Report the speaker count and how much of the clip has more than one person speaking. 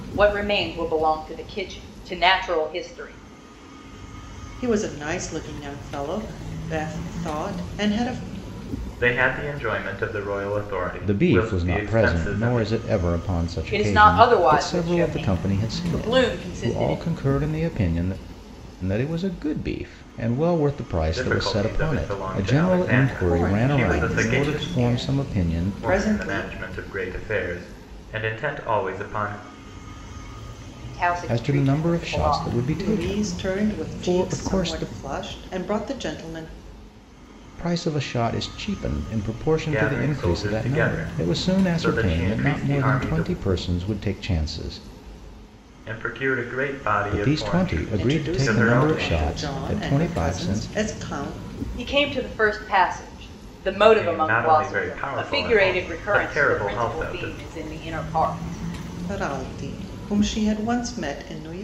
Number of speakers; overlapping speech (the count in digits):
4, about 41%